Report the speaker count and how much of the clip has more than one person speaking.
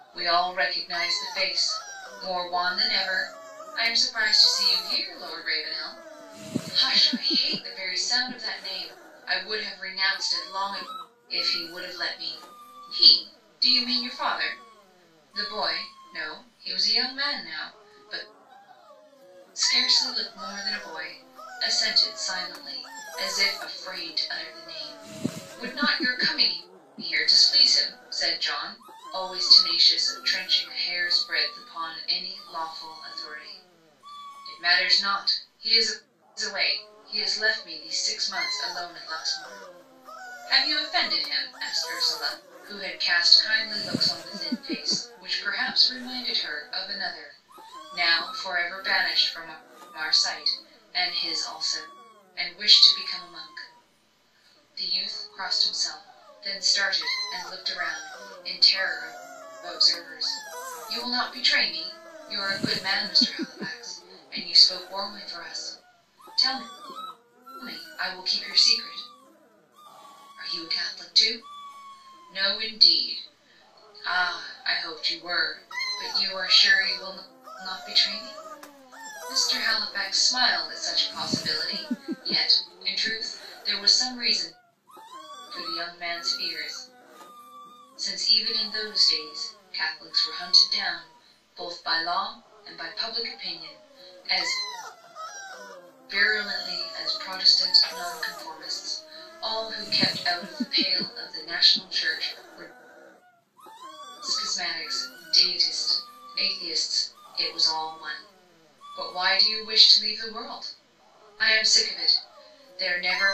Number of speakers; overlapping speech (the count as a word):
one, no overlap